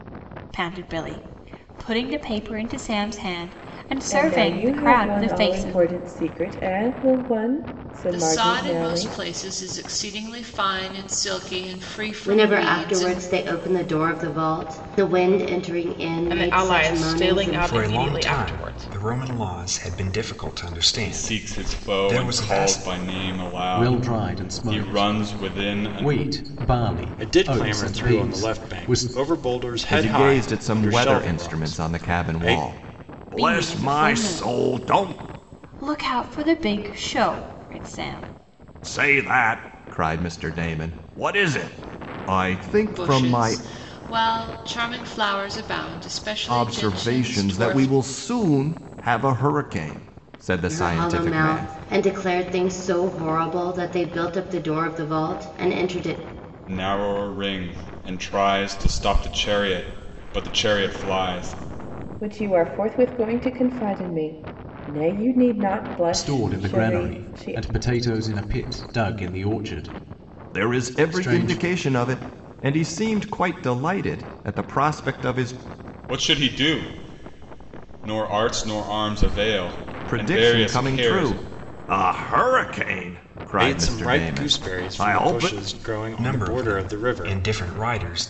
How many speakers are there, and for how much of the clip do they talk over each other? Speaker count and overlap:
10, about 32%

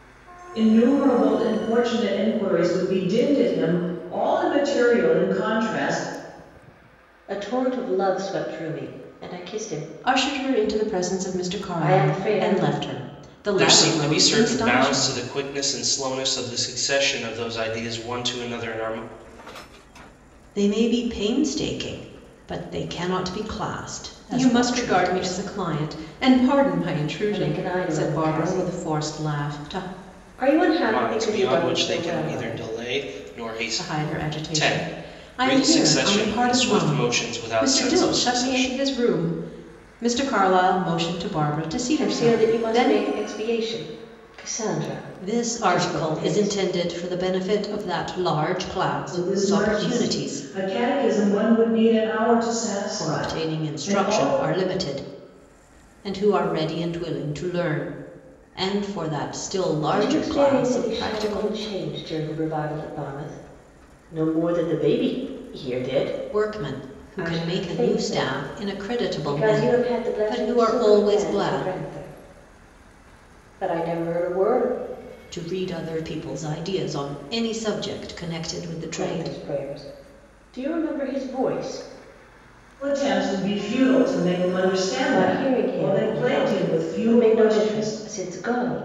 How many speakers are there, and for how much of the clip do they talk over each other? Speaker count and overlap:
5, about 33%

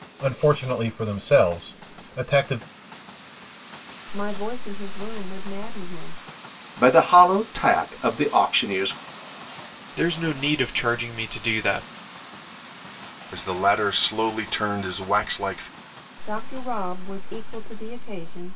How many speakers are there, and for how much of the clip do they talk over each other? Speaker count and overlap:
5, no overlap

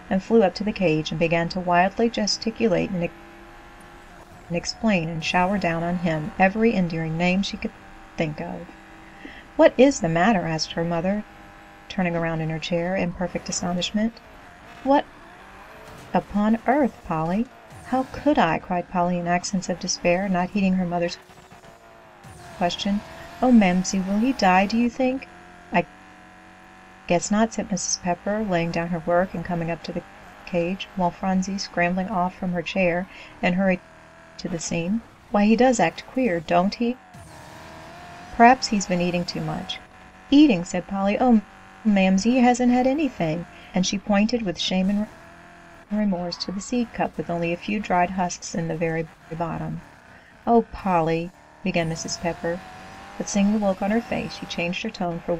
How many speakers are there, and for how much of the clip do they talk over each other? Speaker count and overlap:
1, no overlap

